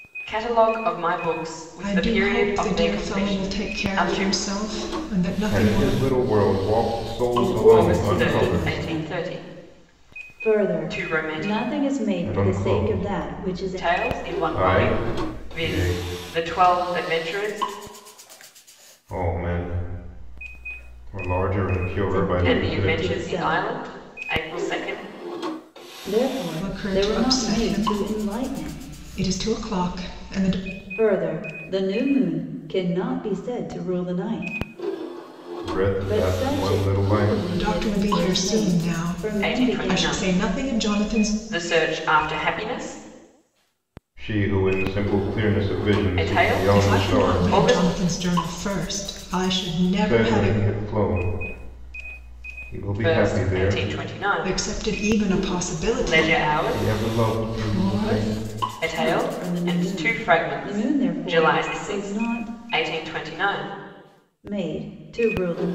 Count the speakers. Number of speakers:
four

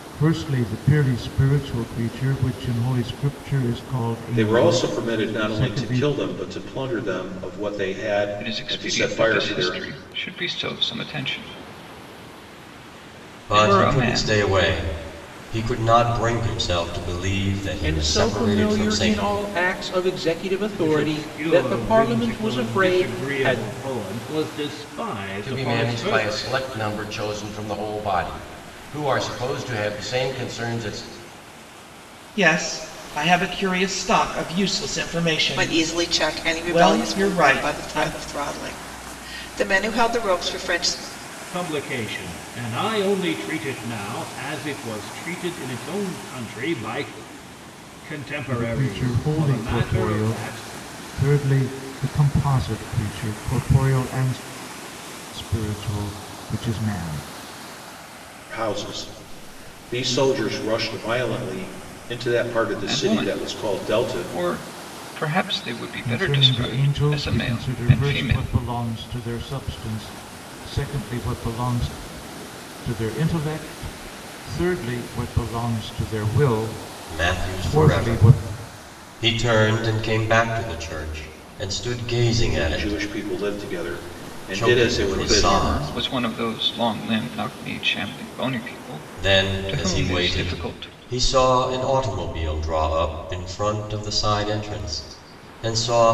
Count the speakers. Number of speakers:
nine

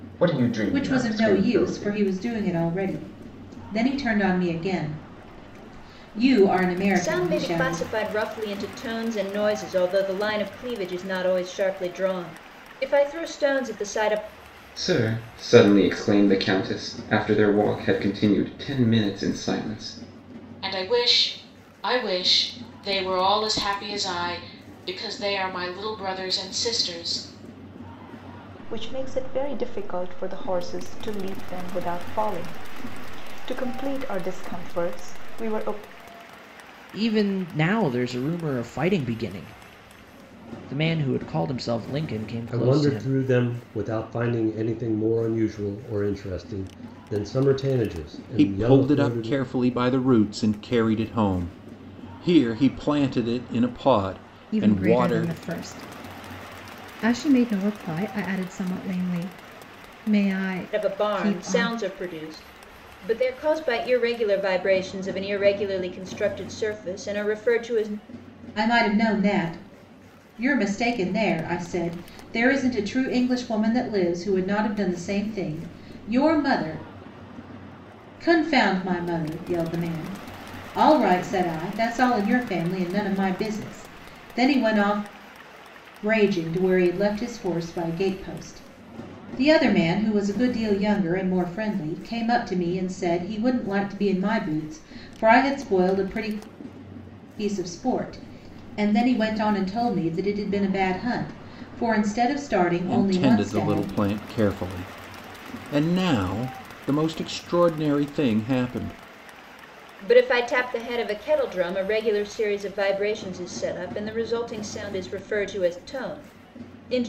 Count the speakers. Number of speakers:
ten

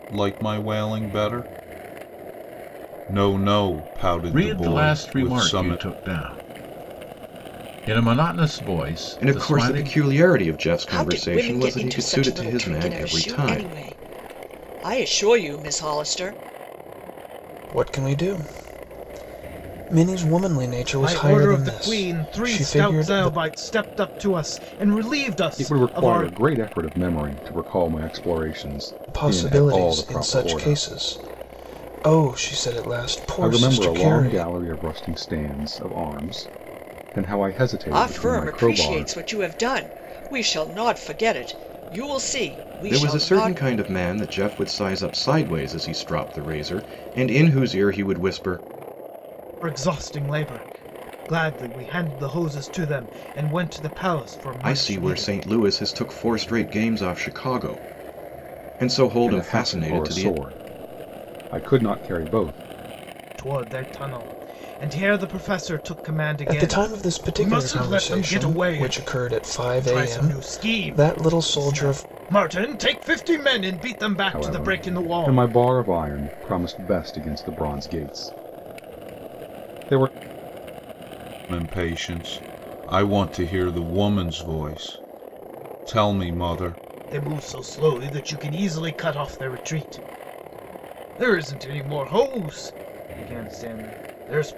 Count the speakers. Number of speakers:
seven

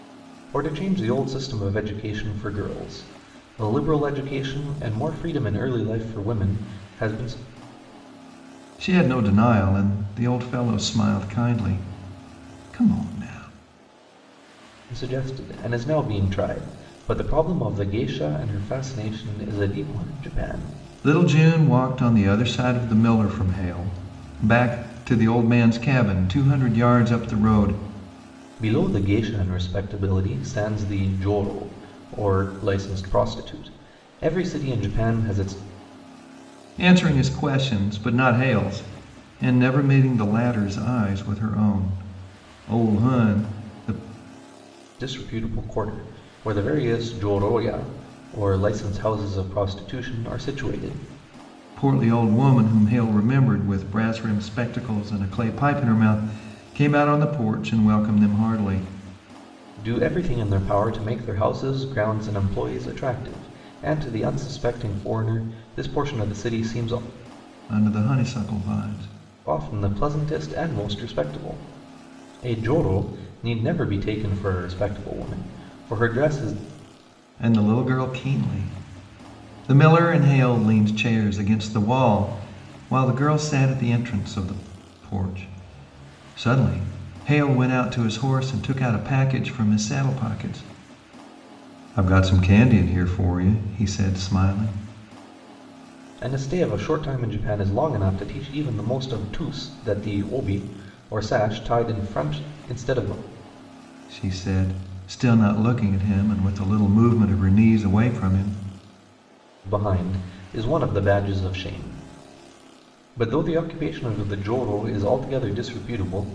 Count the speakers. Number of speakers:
two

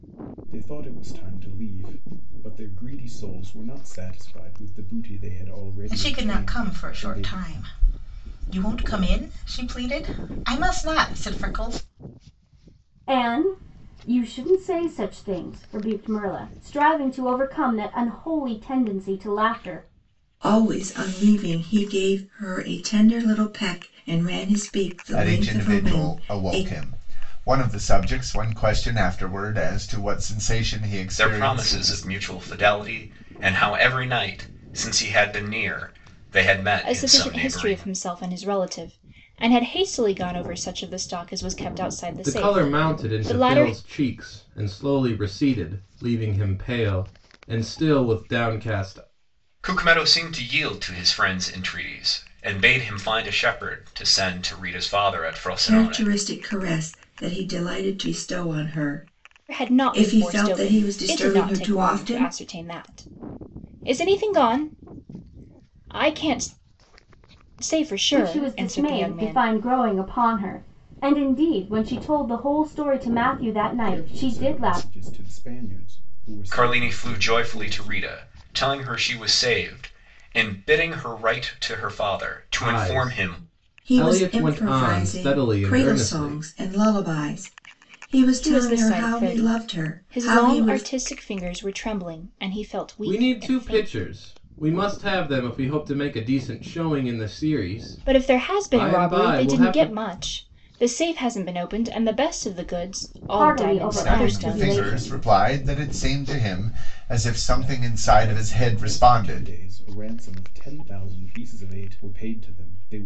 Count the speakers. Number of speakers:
eight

